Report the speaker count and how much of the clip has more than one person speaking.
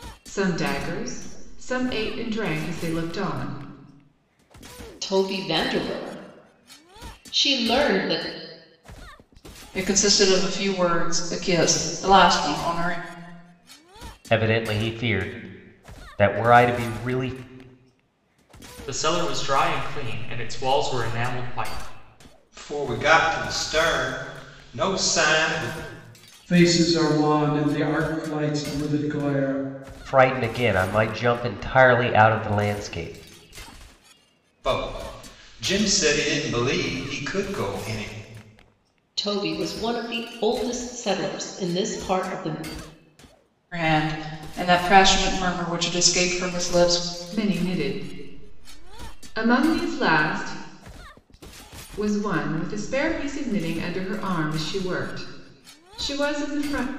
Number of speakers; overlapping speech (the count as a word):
seven, no overlap